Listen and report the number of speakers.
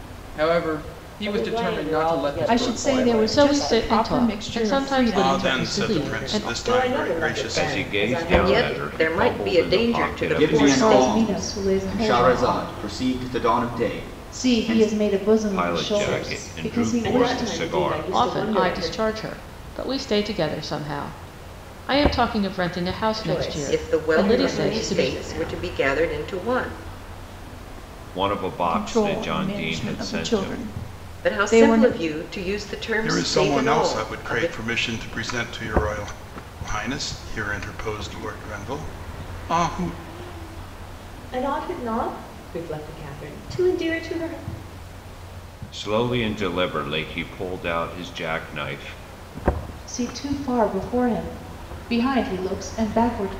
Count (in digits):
10